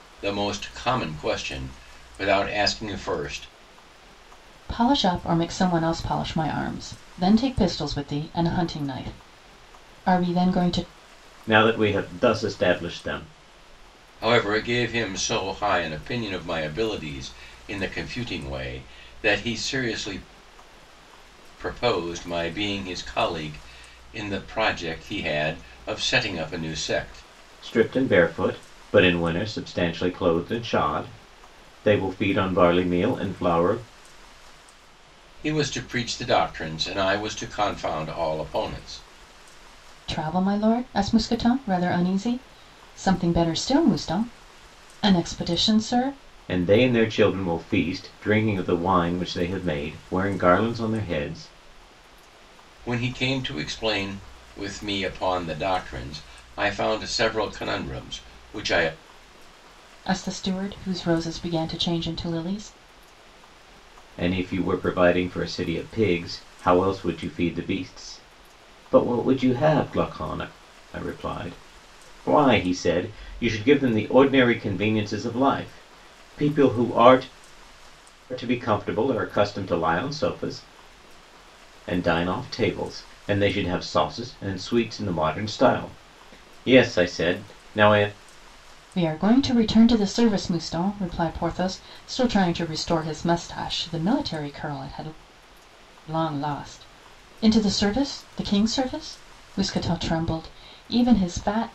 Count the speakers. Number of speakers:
three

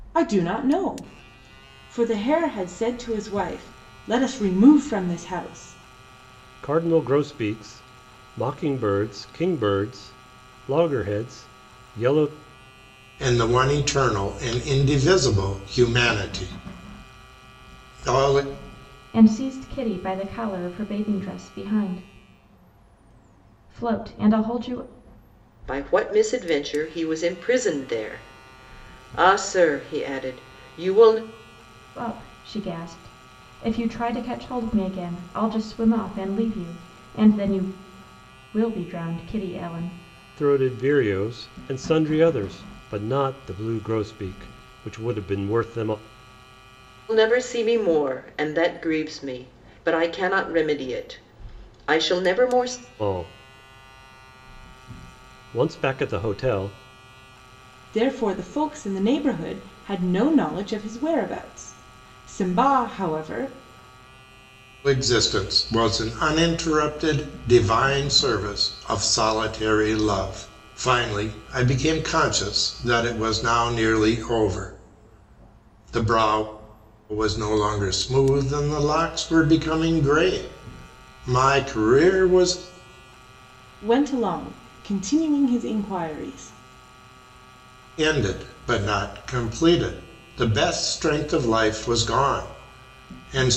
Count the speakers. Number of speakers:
five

